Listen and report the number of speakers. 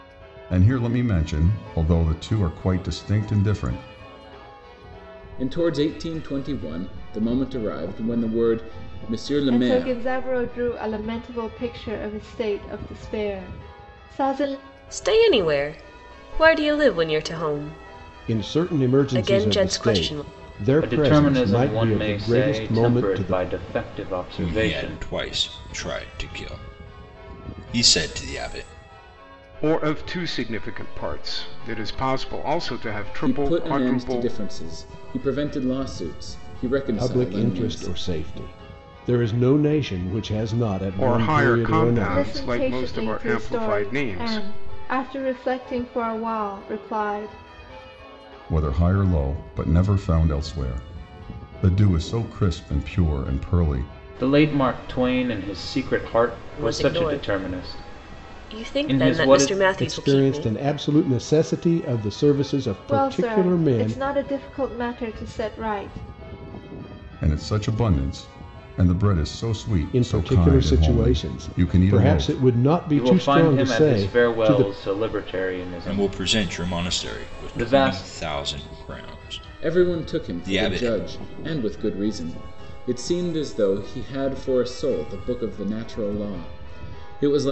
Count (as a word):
eight